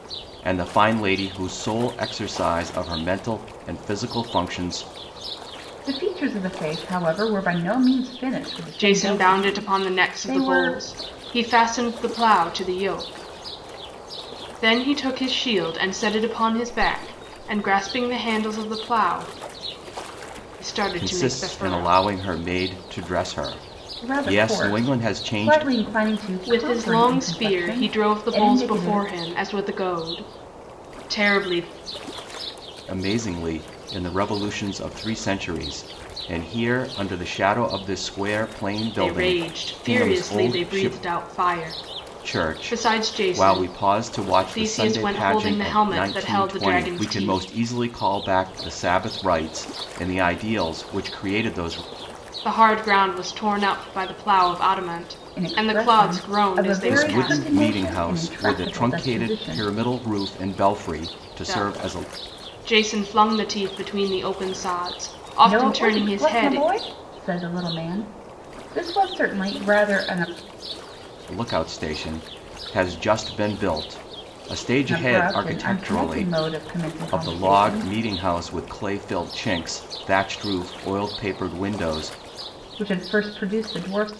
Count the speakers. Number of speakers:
three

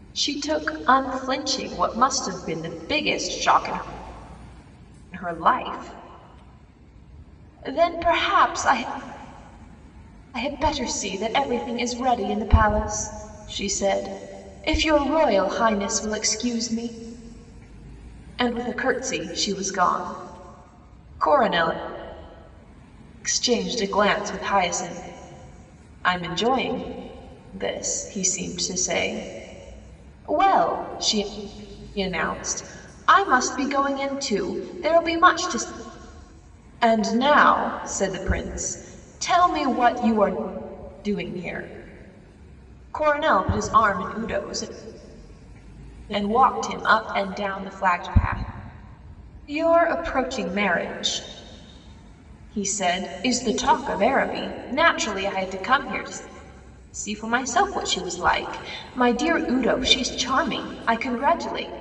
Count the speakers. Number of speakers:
one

